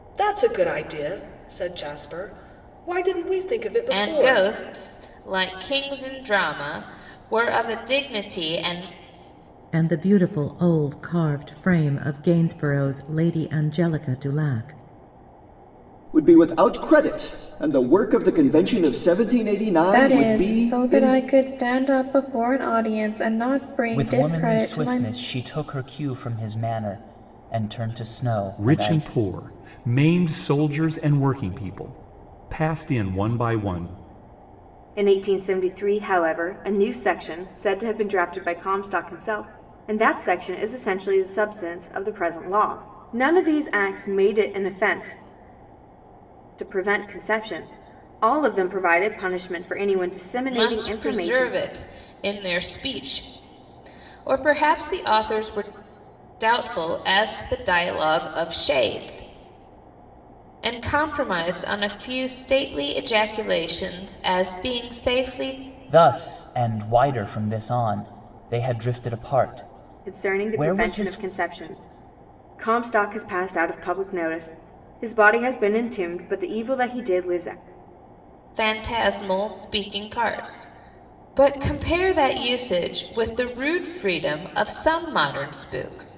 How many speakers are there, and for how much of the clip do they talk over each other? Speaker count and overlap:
8, about 7%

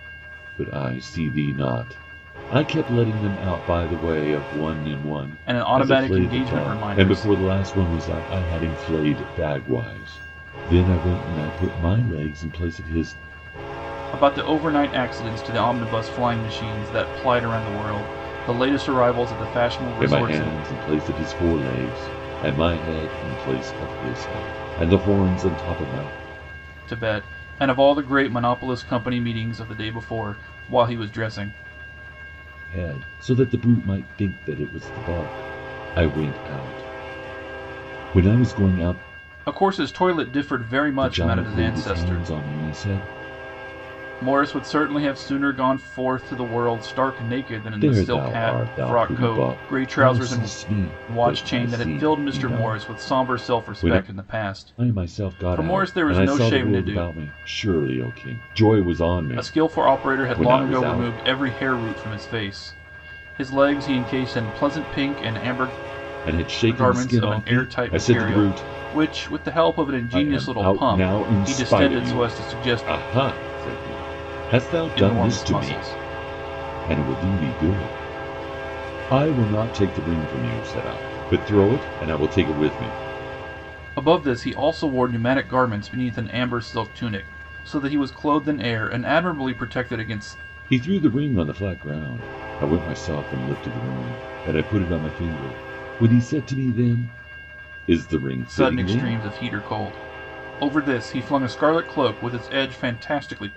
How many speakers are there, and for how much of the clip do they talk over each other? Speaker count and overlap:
2, about 19%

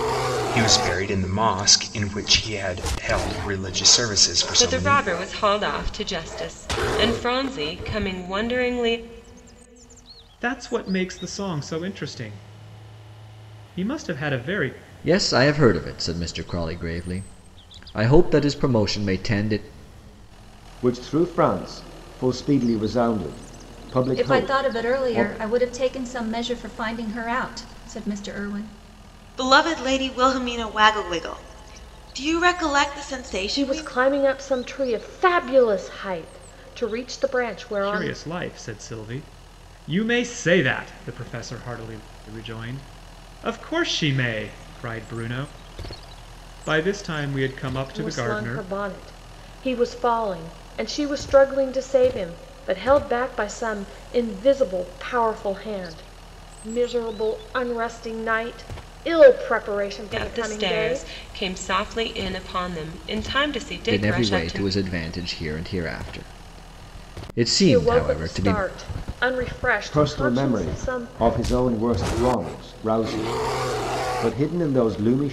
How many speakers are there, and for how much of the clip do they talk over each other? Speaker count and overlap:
8, about 10%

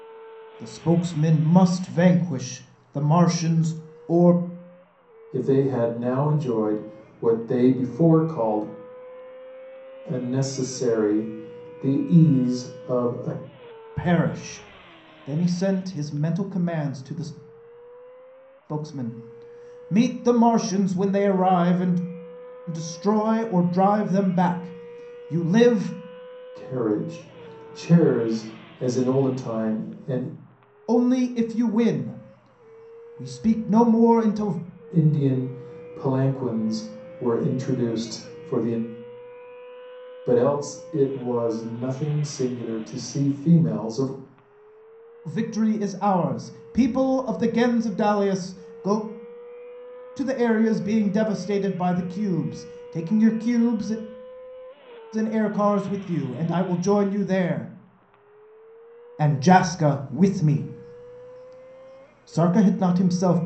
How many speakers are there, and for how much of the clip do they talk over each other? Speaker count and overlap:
2, no overlap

